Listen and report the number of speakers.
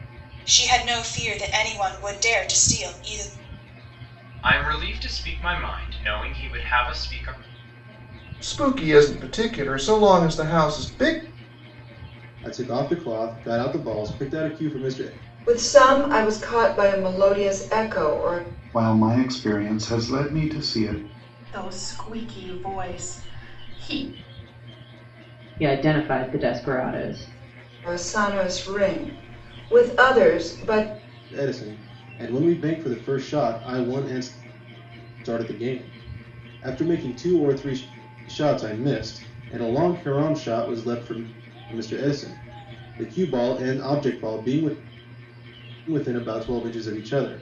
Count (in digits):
8